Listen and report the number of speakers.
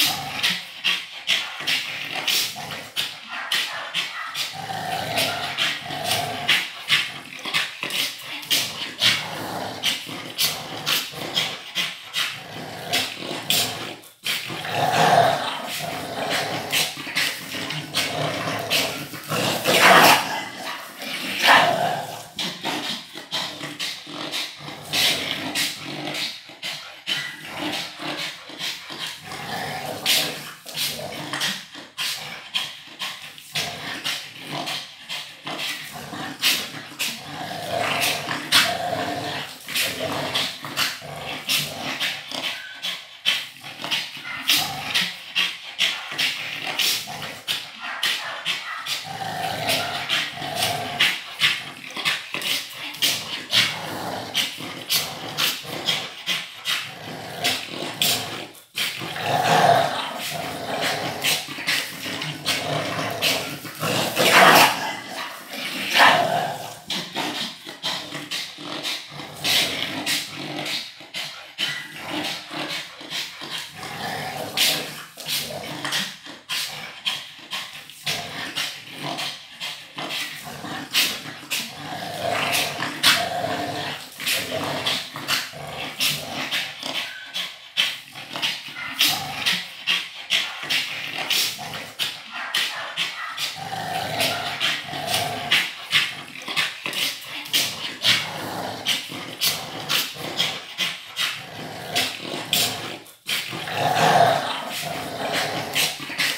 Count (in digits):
0